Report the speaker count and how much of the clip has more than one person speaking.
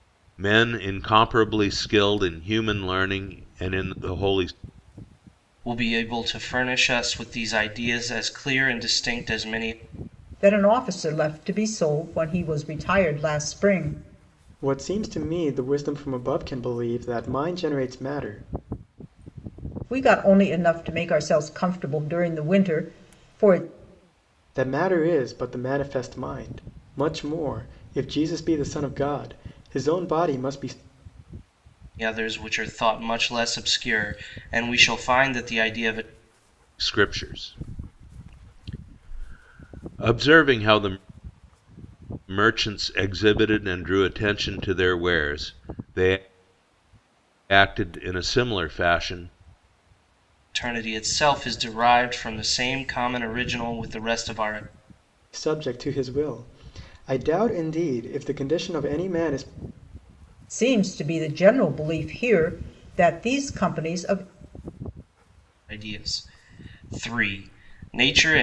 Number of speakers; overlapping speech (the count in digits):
4, no overlap